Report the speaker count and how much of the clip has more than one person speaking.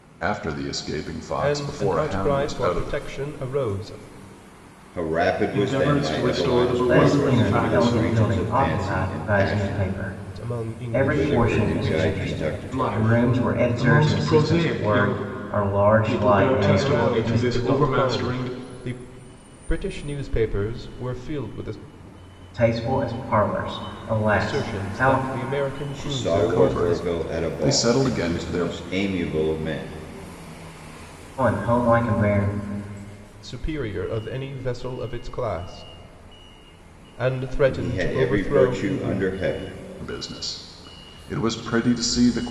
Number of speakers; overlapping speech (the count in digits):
5, about 44%